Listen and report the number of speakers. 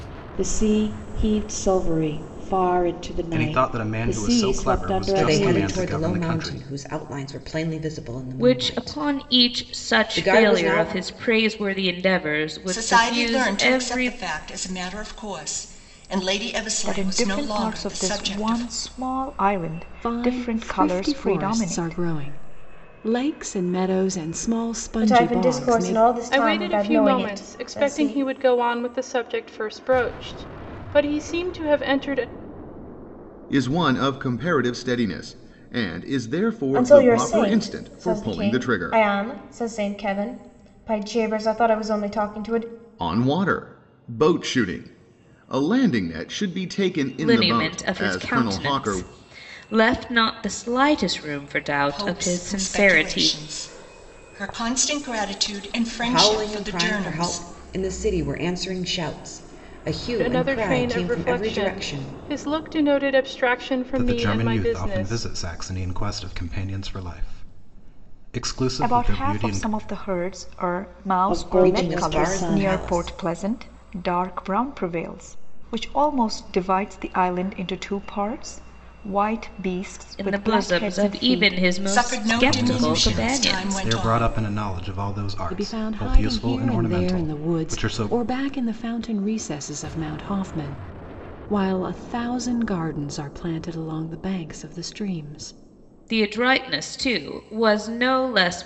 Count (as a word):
ten